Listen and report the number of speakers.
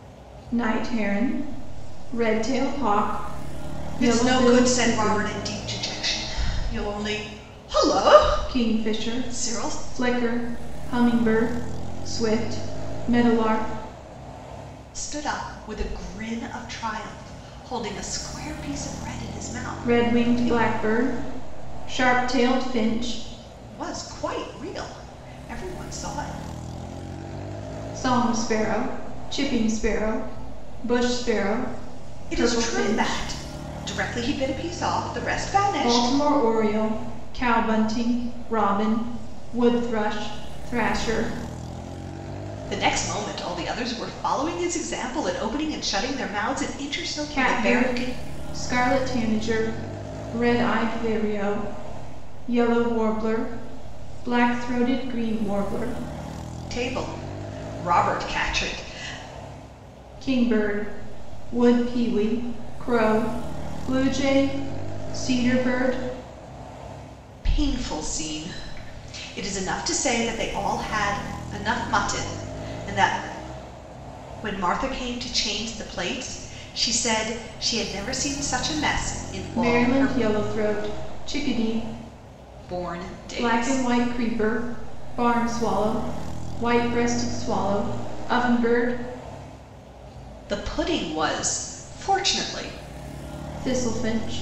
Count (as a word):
two